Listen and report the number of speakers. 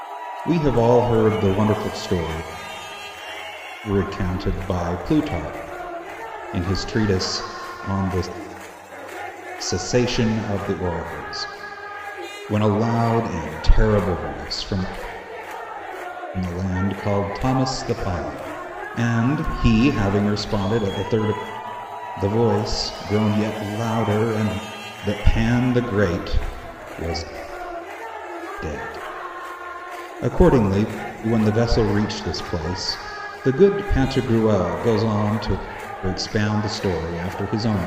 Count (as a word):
one